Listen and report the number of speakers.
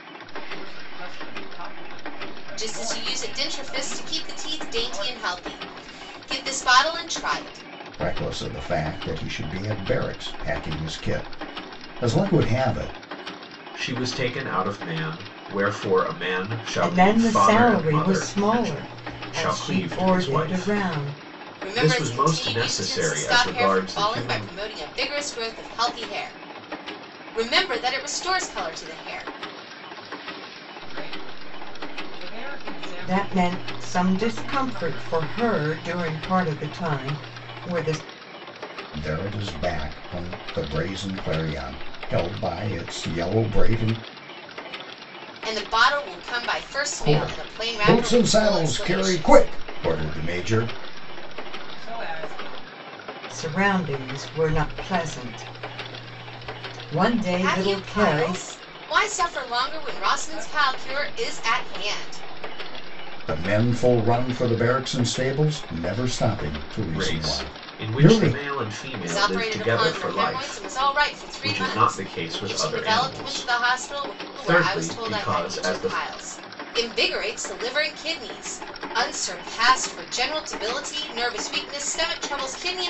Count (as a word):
five